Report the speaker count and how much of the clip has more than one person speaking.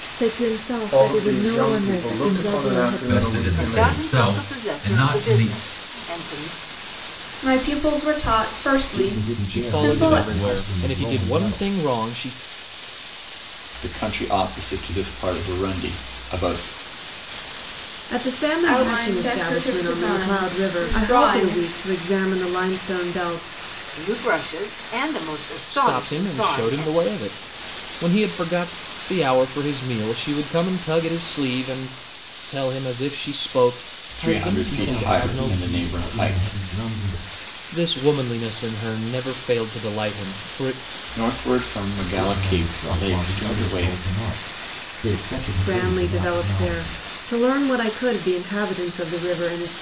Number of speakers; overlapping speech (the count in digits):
9, about 36%